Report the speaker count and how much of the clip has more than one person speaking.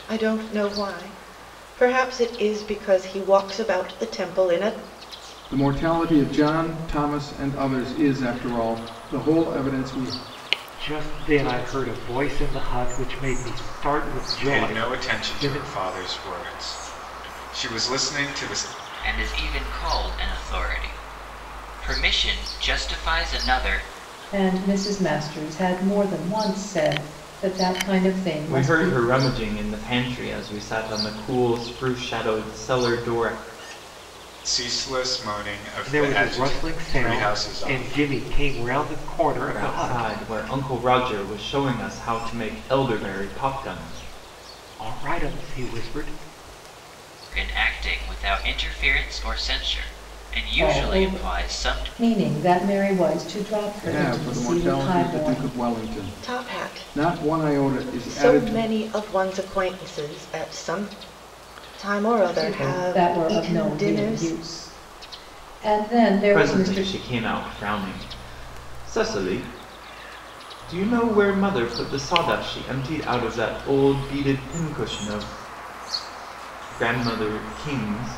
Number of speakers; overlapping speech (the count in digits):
7, about 16%